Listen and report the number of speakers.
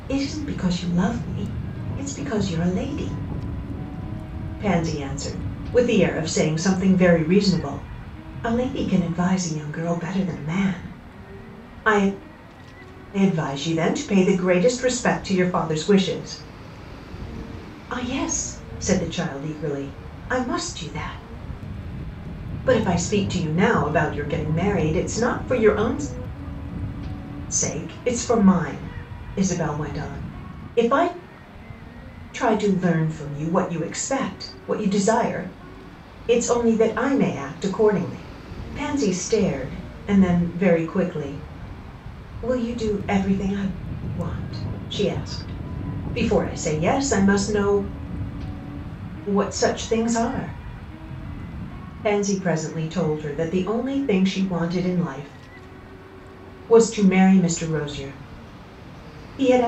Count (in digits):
1